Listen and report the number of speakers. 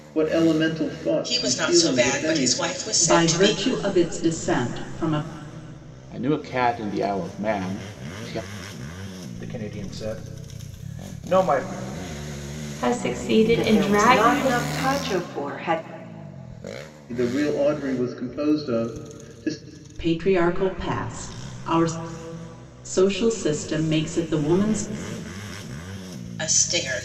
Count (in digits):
7